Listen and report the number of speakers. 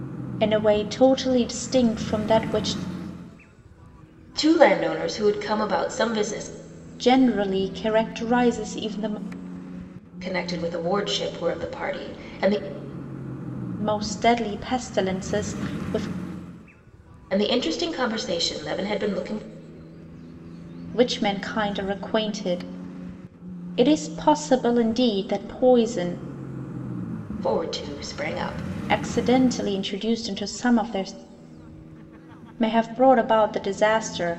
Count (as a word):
two